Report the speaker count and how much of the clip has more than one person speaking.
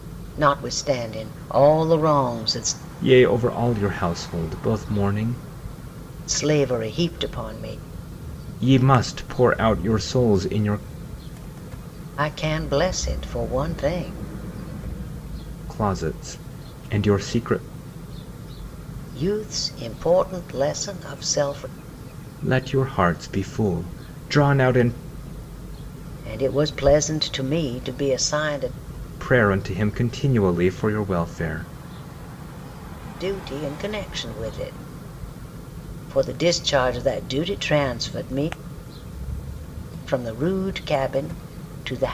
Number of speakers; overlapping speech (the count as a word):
two, no overlap